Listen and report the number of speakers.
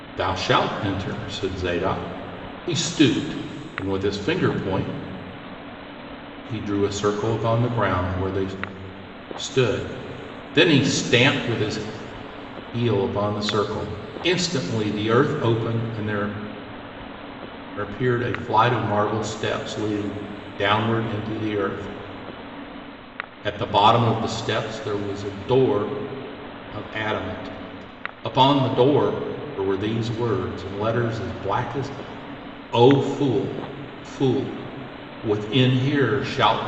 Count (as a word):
one